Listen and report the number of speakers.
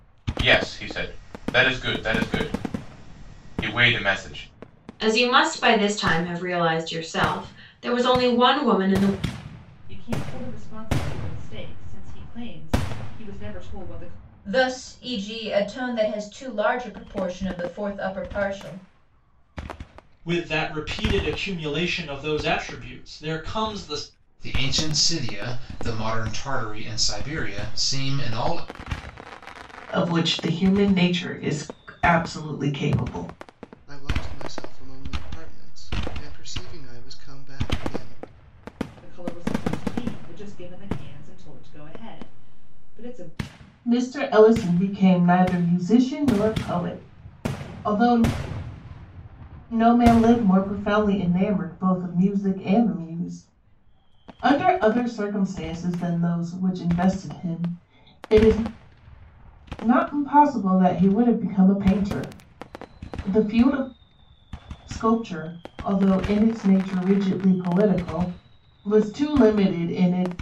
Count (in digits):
8